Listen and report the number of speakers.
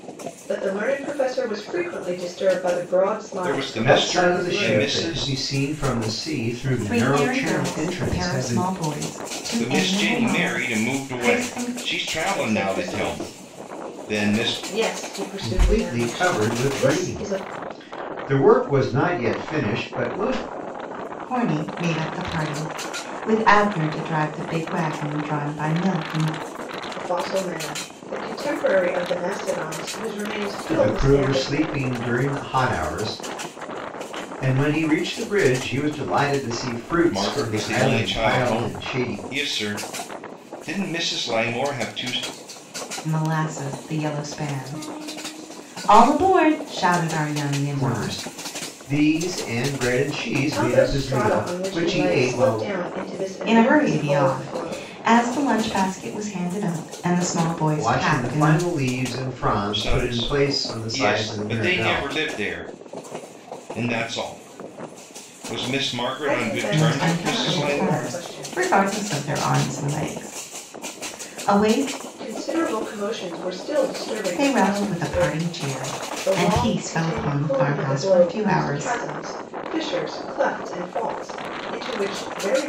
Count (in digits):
4